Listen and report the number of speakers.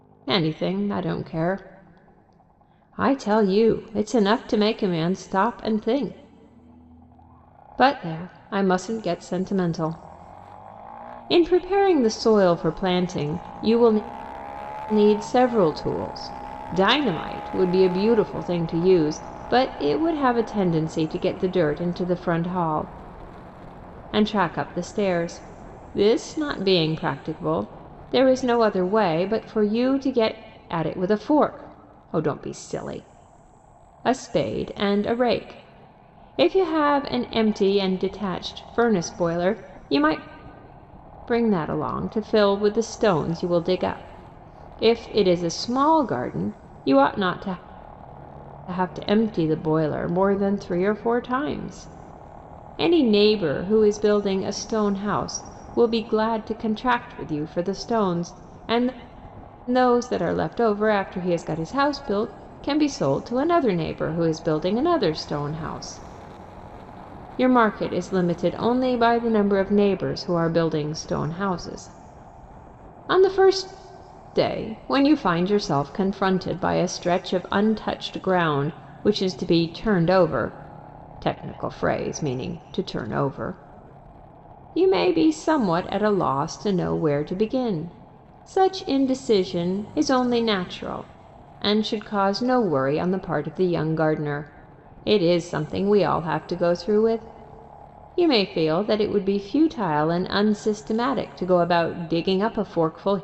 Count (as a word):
one